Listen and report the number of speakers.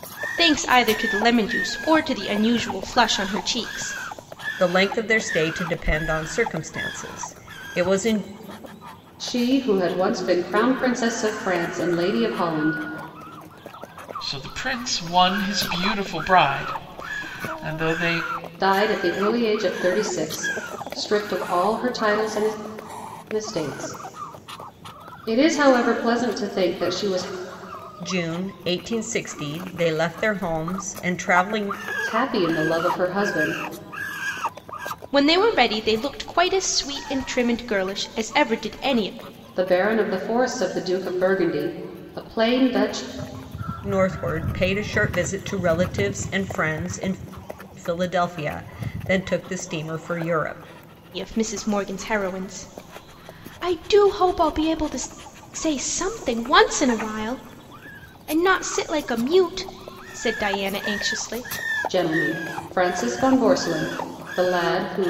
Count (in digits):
4